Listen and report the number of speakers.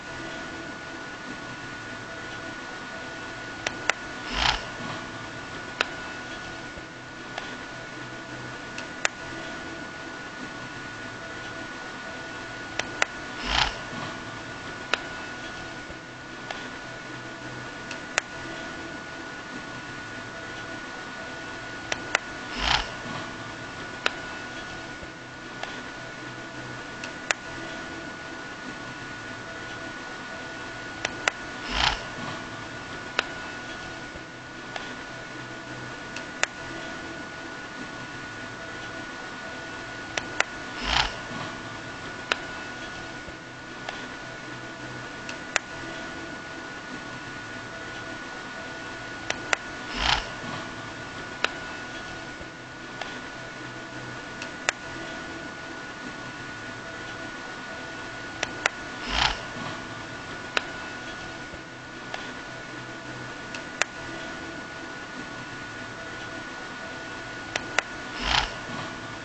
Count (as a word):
zero